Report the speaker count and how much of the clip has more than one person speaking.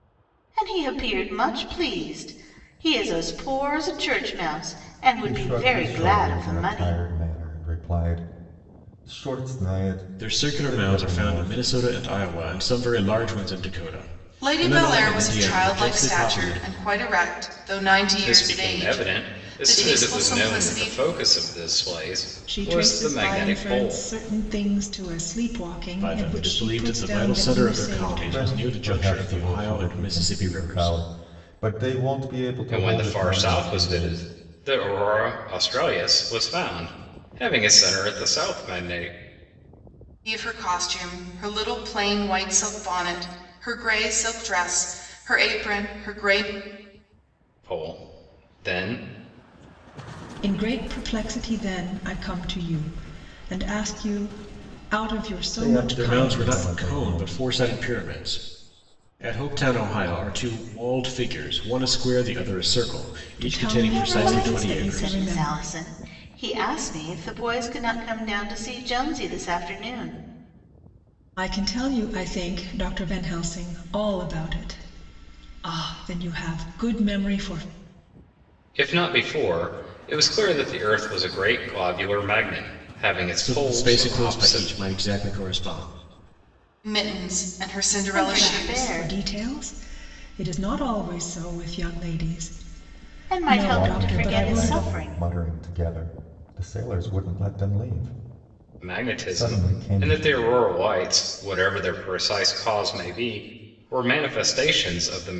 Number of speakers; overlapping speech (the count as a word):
six, about 25%